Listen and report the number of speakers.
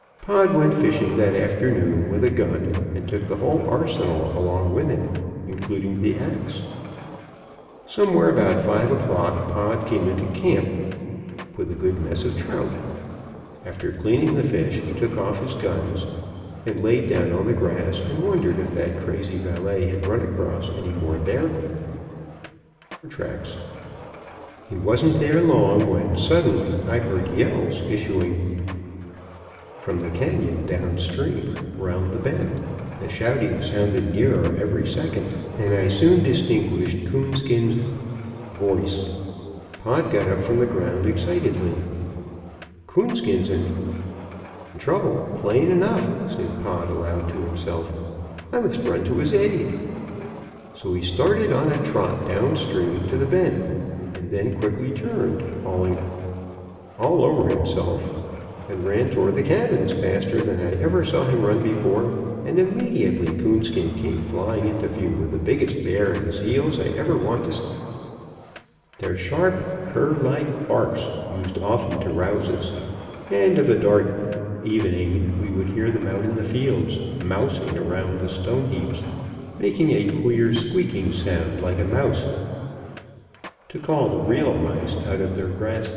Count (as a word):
one